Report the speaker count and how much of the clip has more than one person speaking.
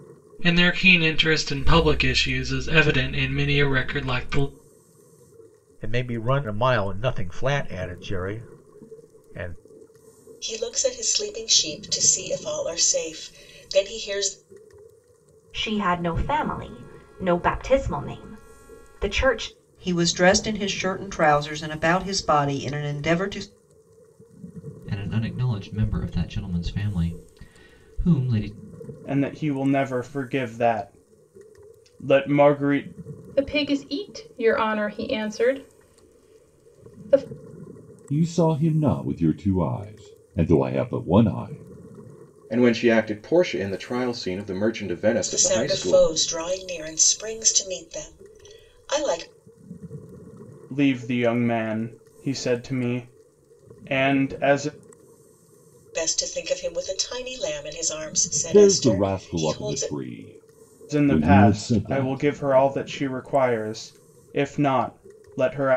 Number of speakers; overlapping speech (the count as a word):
ten, about 6%